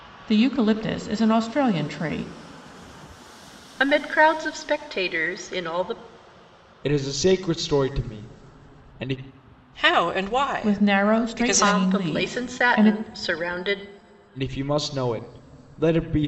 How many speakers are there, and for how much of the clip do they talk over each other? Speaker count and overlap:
4, about 15%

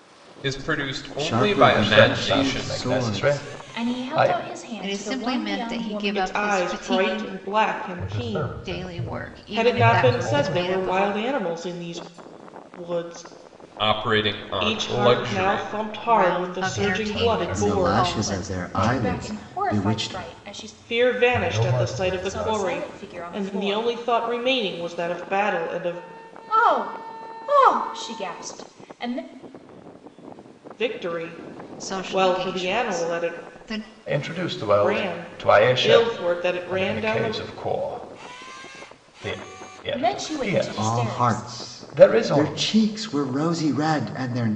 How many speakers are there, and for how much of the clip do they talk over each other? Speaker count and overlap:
7, about 56%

